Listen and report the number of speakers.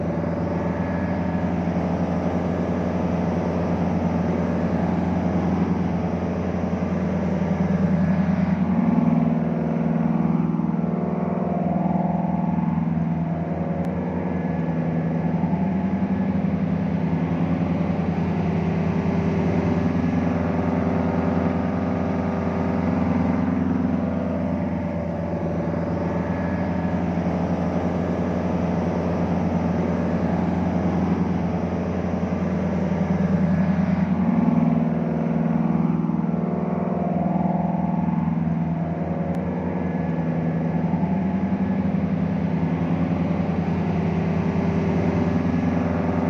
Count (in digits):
0